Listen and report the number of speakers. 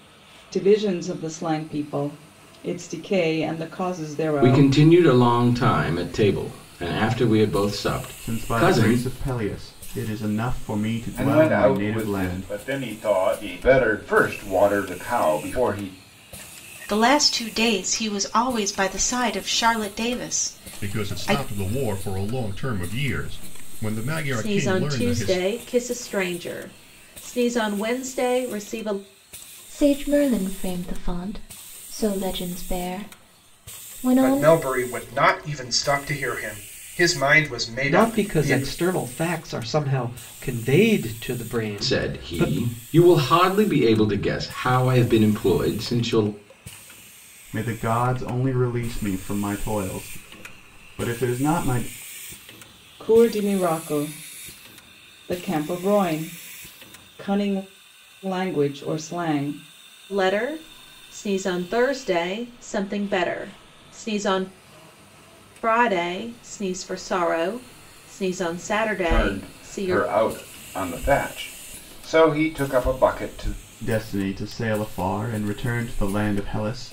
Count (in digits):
10